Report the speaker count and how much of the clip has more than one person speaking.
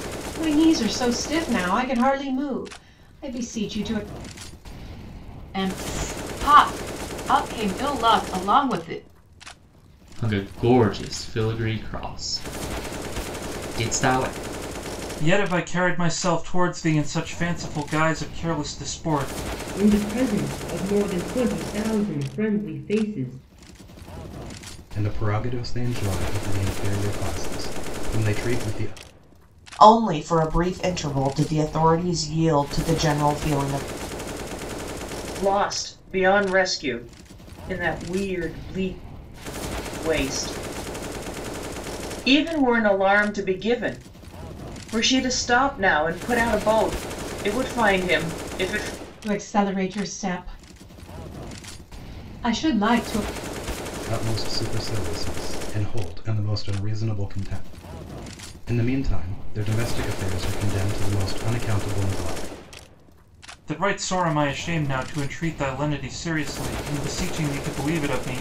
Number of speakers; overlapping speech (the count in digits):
8, no overlap